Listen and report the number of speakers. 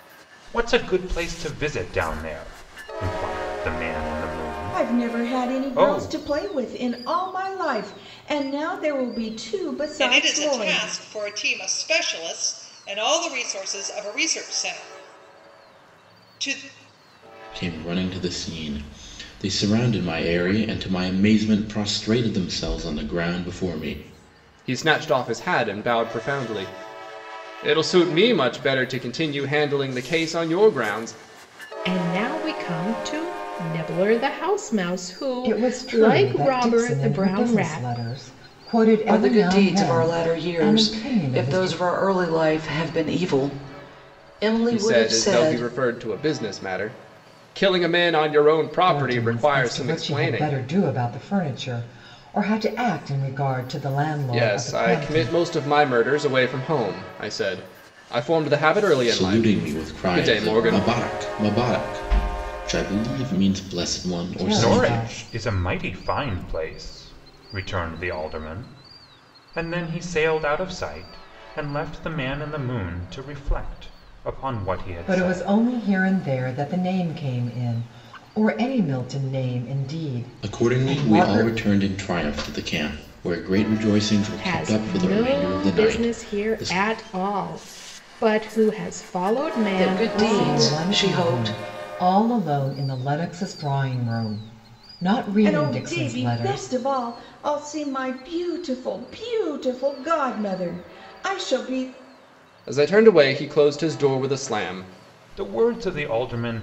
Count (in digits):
8